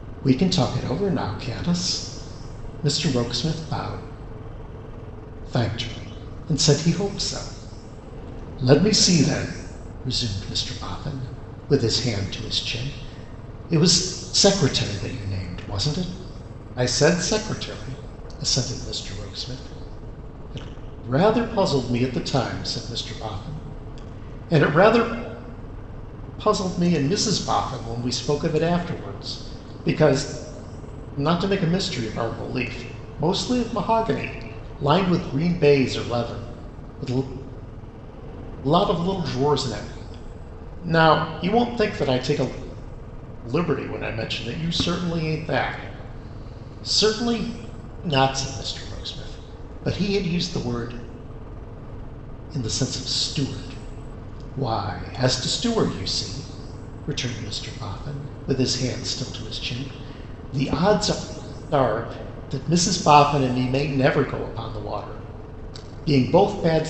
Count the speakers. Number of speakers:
one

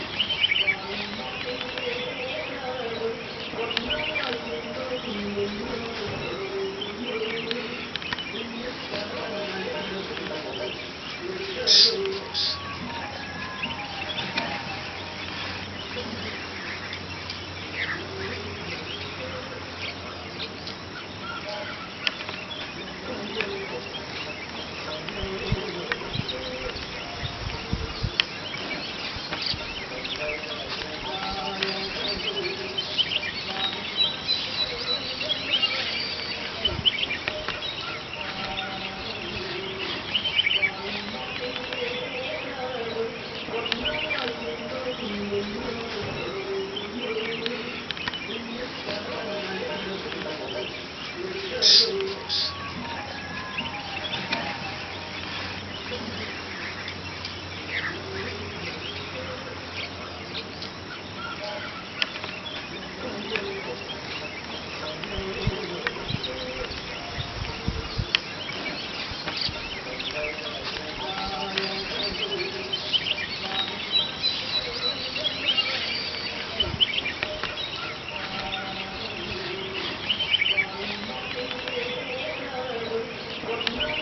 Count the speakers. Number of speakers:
zero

